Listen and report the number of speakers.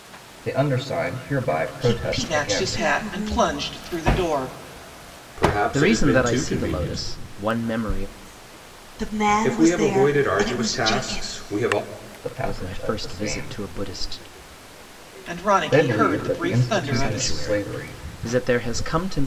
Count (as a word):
five